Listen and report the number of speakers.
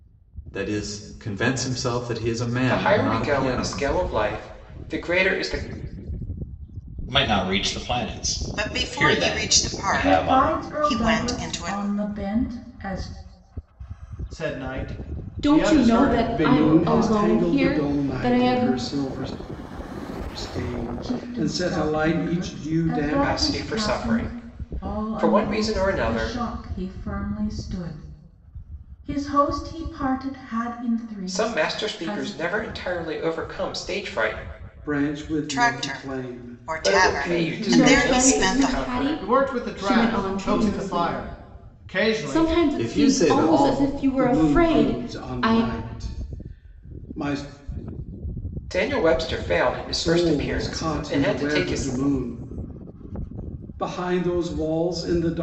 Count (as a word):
eight